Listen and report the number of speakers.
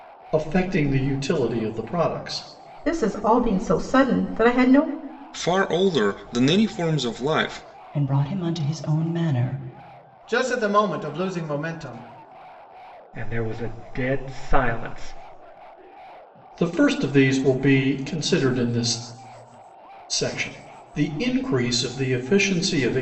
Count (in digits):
6